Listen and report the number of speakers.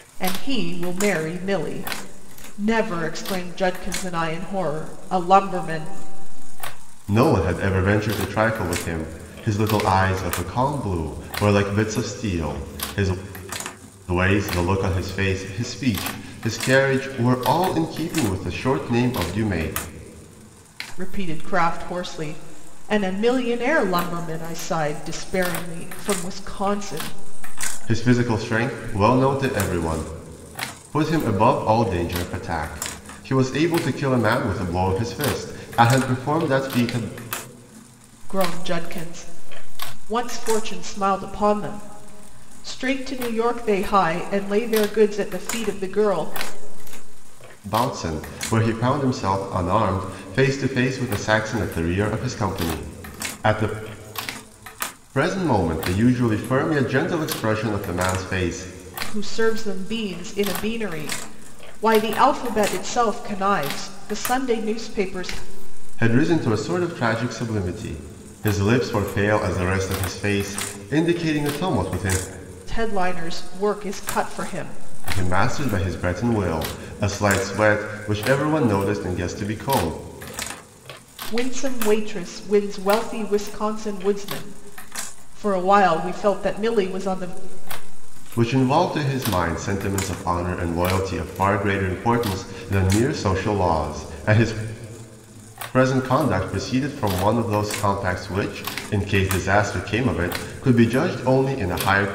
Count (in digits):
2